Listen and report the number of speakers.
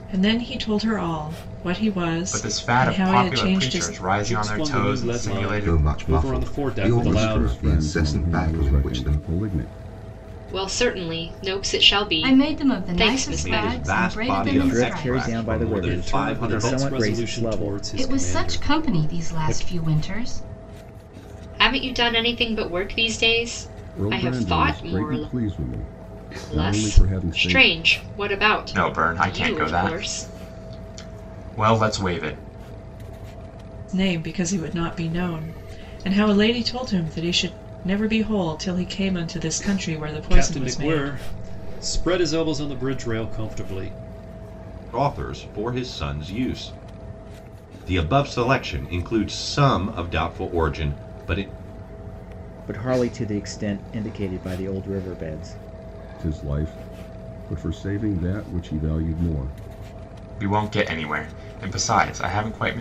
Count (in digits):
9